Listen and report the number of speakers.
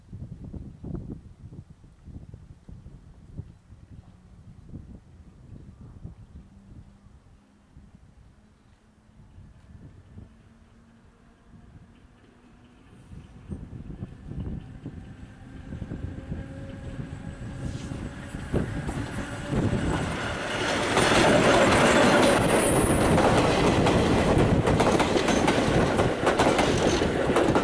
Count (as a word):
zero